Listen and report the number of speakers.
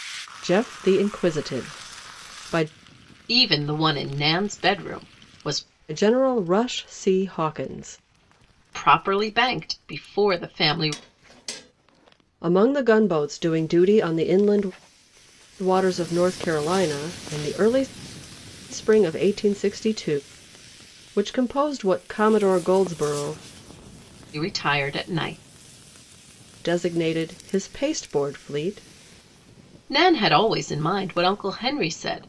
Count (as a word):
two